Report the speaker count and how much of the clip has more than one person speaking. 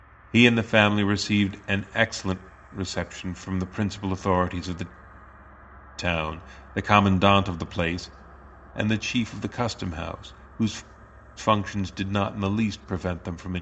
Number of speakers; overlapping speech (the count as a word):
one, no overlap